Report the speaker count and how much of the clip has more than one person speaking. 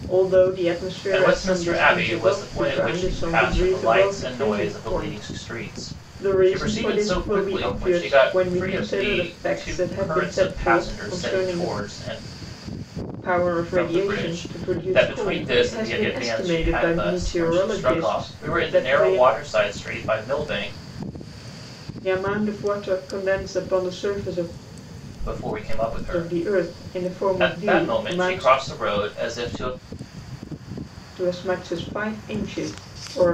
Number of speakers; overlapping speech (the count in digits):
2, about 56%